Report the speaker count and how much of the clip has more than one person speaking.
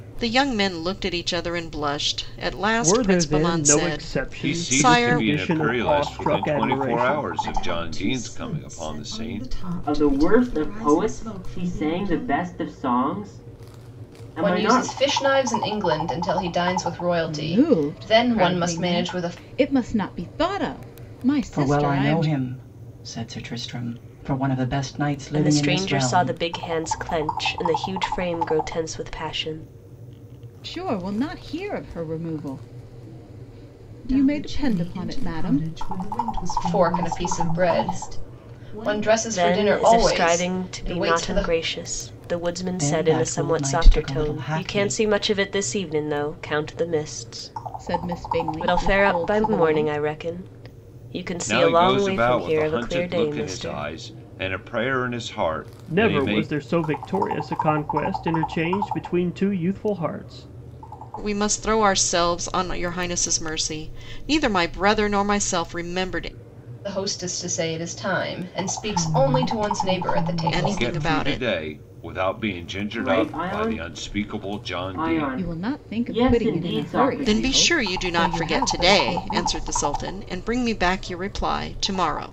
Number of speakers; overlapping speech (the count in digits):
9, about 45%